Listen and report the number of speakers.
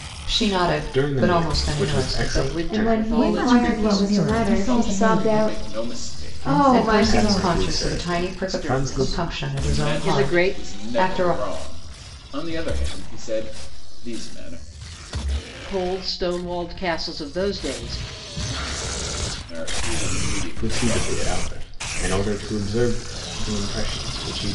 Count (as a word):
six